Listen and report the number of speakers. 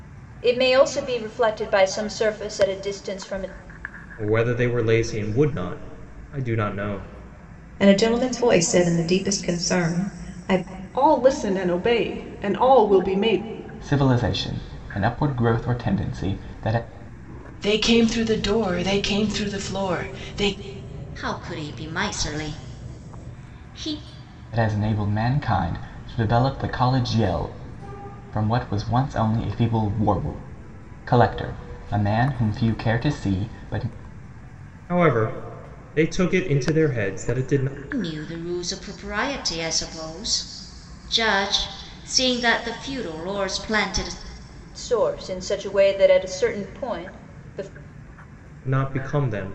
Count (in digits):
7